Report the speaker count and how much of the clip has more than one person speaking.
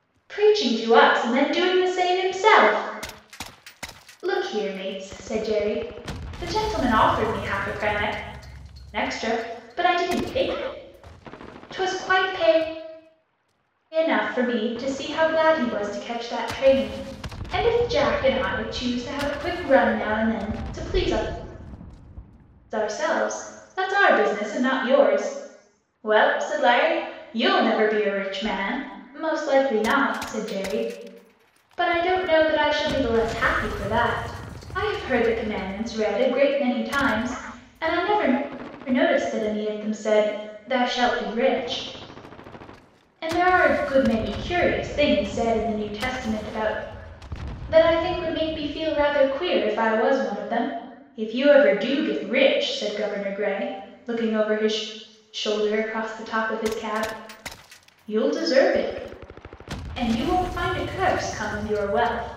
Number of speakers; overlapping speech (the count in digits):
1, no overlap